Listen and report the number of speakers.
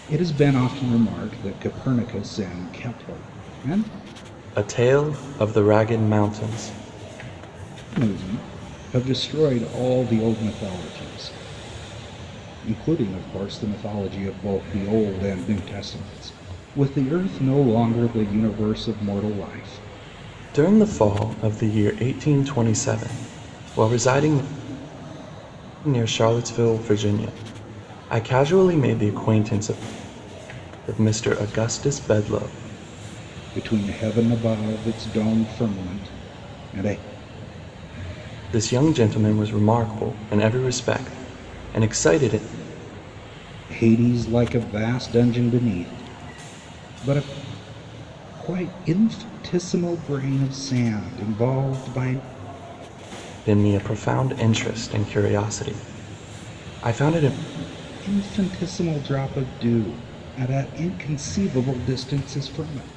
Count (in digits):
2